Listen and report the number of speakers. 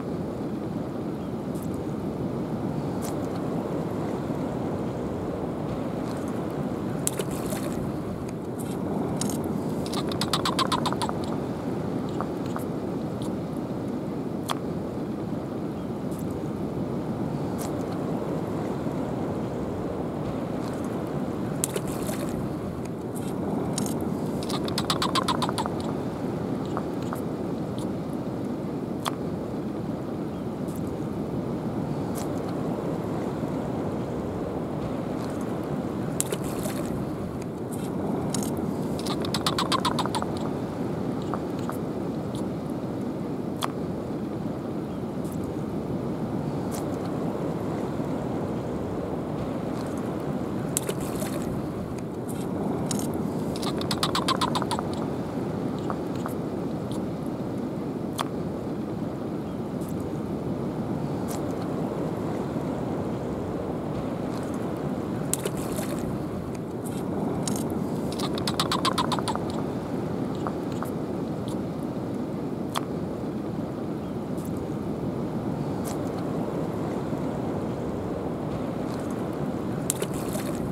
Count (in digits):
0